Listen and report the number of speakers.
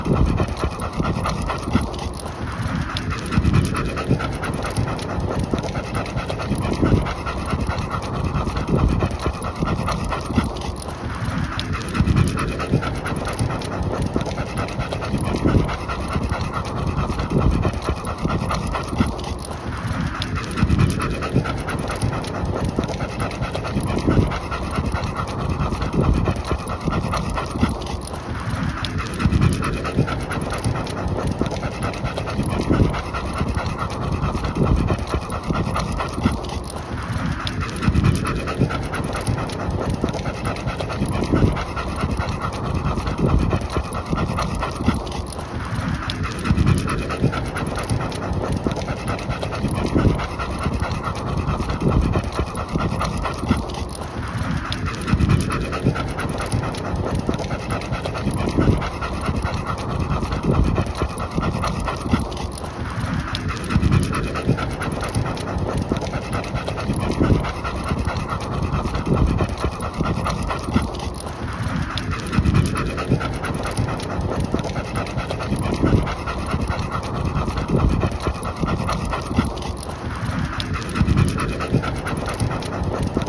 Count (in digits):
0